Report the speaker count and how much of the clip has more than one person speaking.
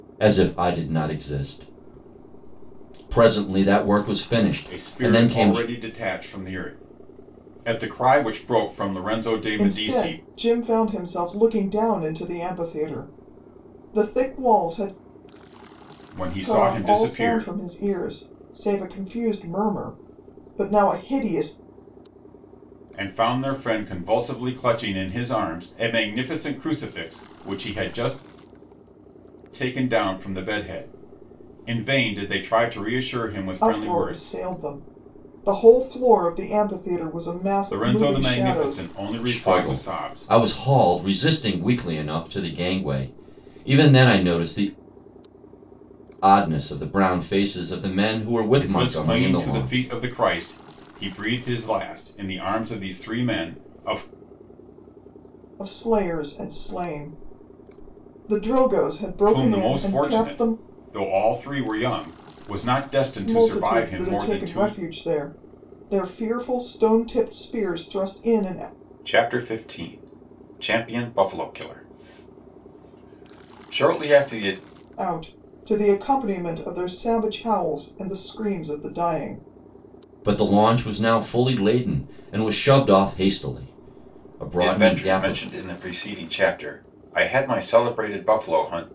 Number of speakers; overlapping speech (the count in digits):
3, about 12%